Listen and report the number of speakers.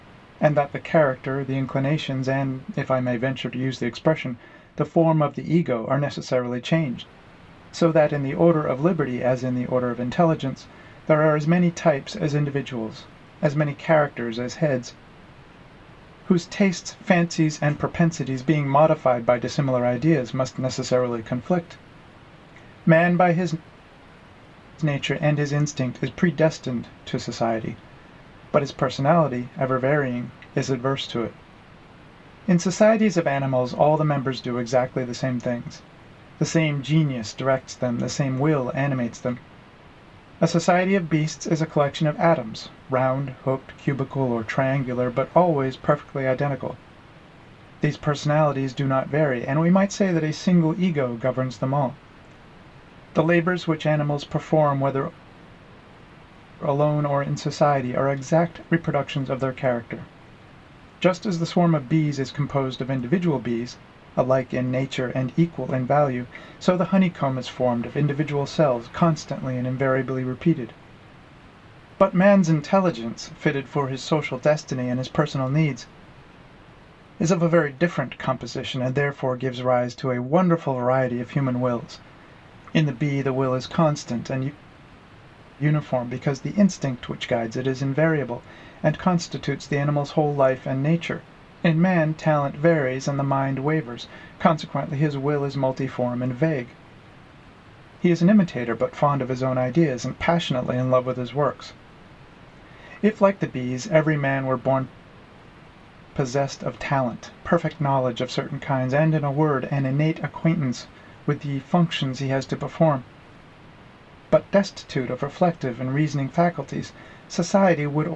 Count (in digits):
1